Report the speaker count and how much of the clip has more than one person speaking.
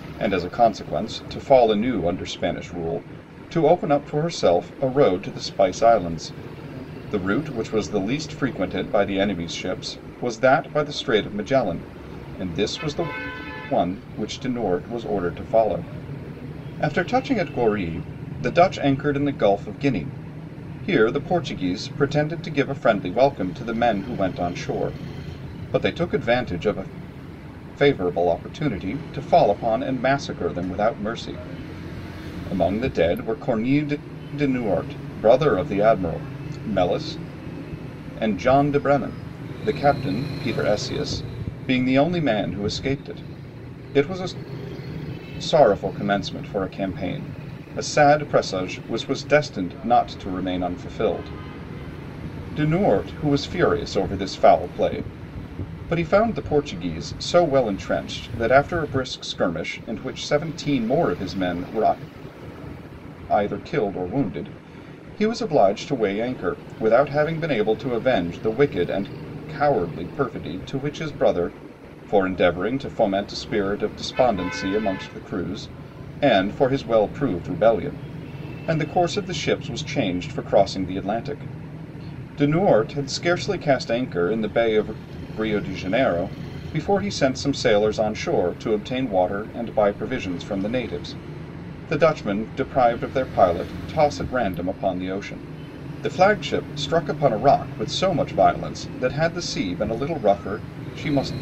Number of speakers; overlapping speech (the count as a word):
one, no overlap